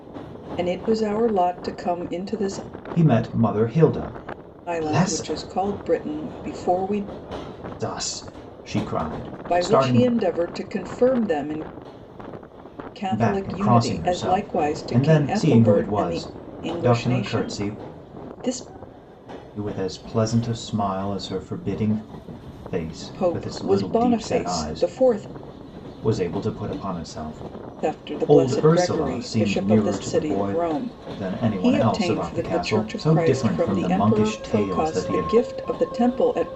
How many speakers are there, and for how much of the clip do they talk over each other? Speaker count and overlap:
two, about 38%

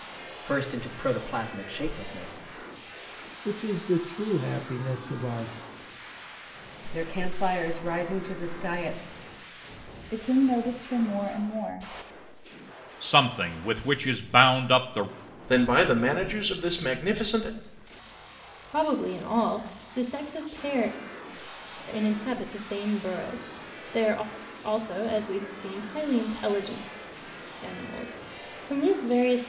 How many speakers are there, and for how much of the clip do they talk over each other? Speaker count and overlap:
seven, no overlap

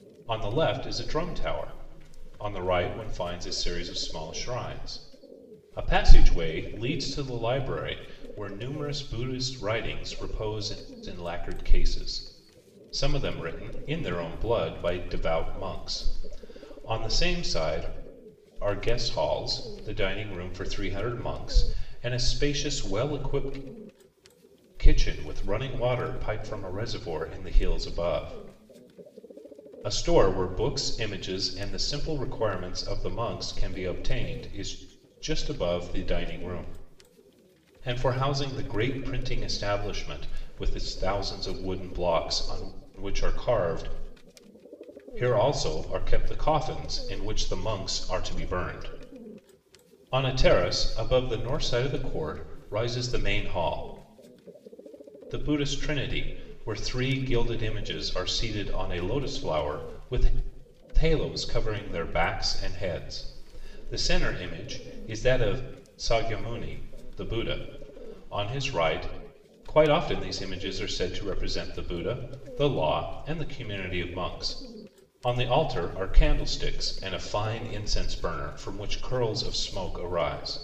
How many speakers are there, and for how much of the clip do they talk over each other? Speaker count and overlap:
one, no overlap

